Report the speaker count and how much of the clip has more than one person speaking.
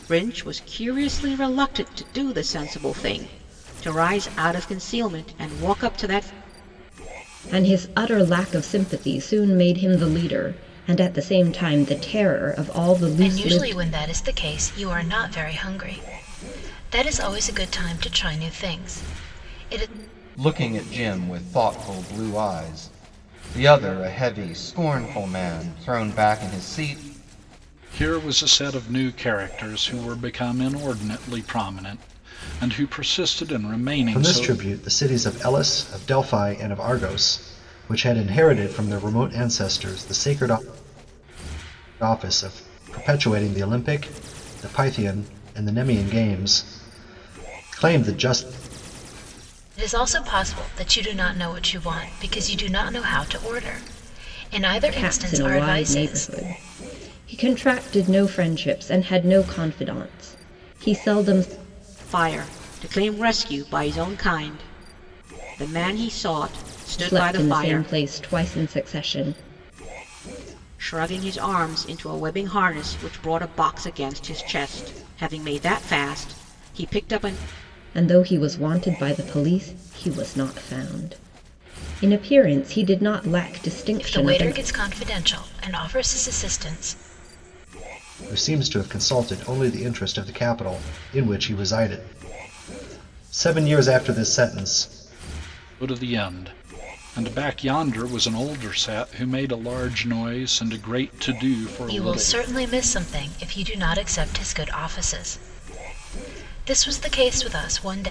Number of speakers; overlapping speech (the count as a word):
six, about 4%